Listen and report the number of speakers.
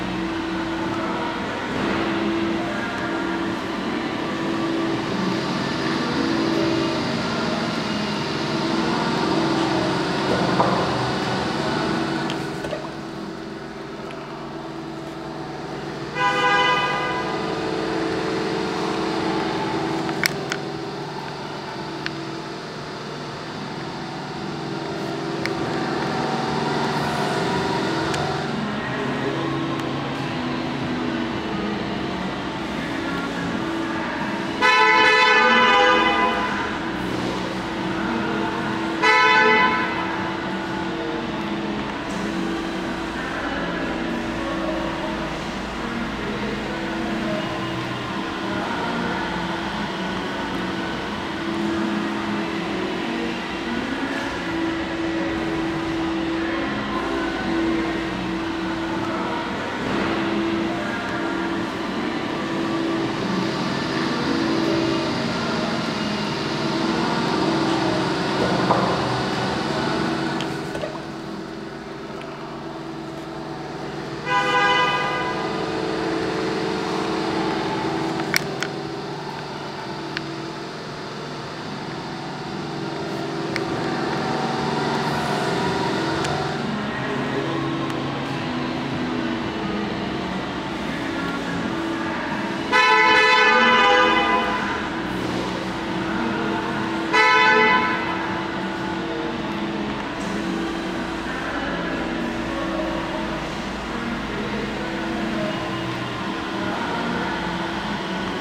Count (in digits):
0